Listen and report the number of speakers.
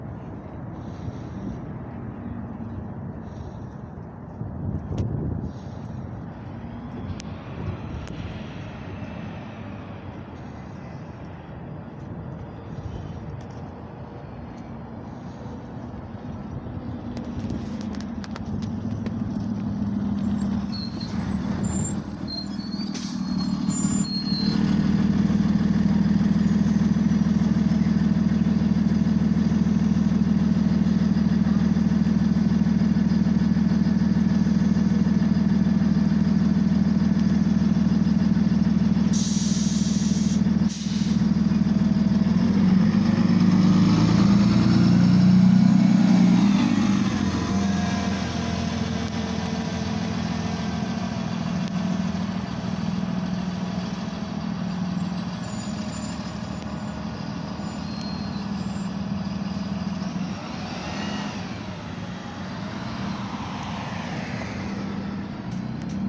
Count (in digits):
0